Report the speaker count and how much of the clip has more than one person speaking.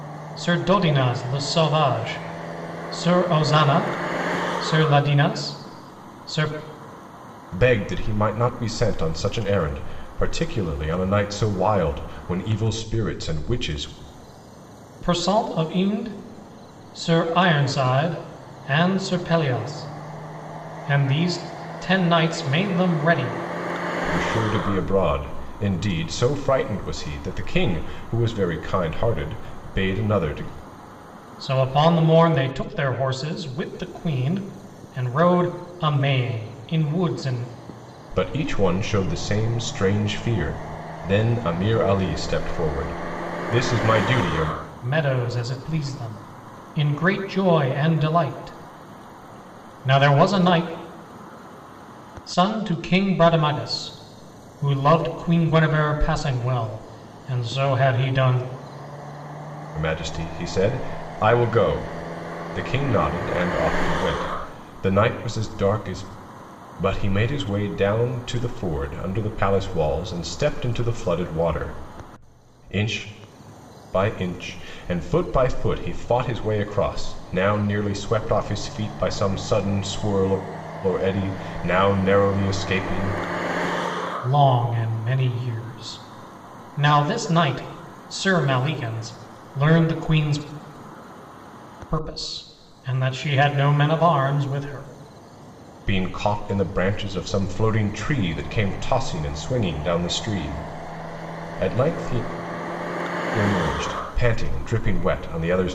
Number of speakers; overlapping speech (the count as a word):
two, no overlap